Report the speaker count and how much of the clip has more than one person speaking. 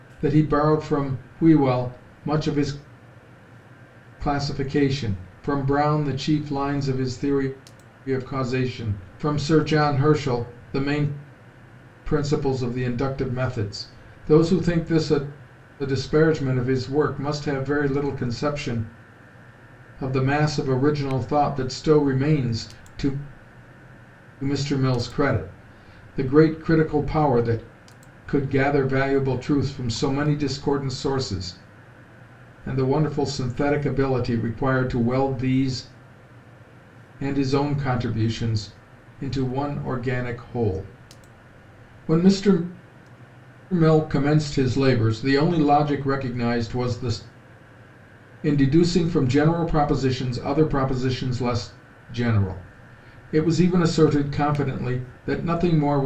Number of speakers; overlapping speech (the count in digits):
1, no overlap